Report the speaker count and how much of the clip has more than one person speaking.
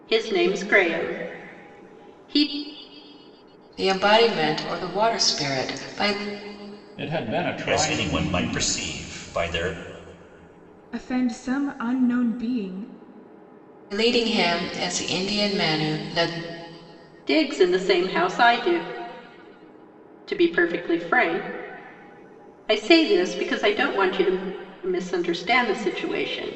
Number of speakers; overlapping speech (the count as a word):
five, about 4%